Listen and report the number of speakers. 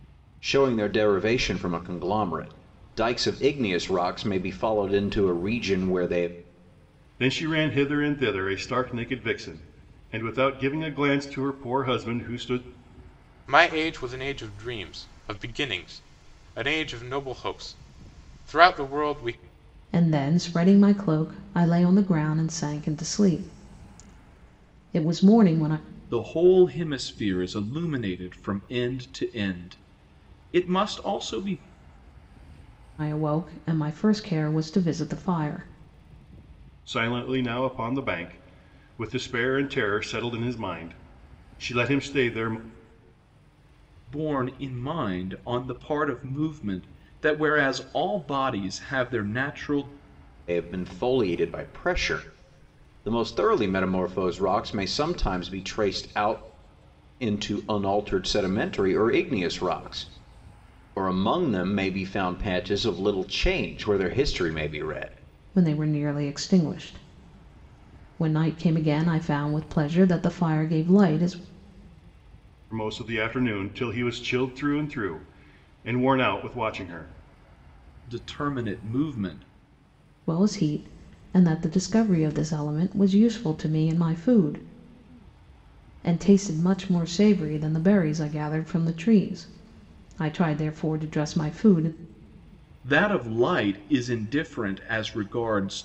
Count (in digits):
5